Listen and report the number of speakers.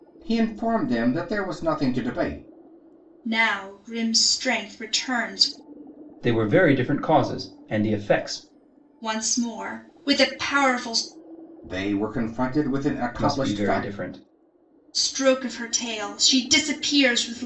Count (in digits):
3